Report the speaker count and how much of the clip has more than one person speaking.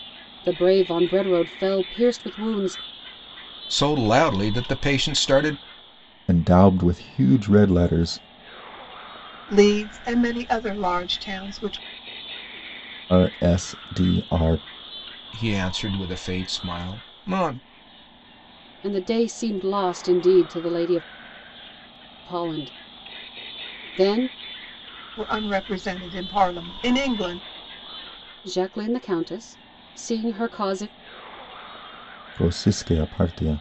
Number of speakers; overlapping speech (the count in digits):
4, no overlap